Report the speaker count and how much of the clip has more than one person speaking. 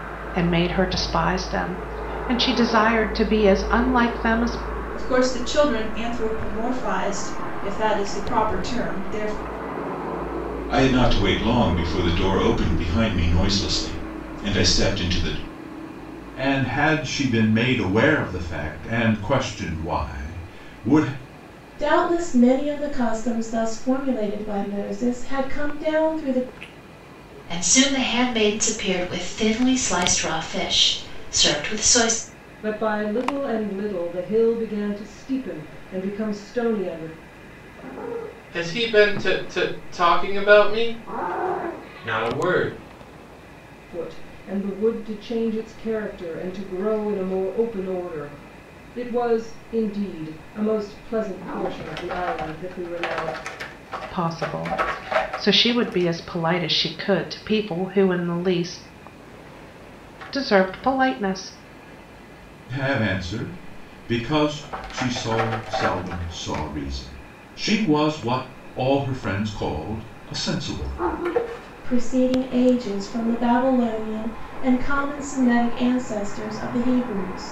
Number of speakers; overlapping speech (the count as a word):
eight, no overlap